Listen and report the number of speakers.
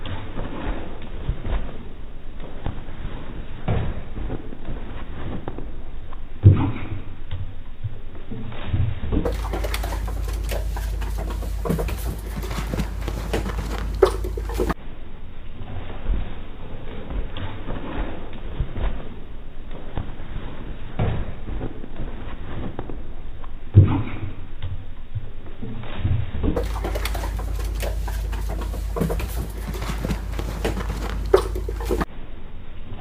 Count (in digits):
0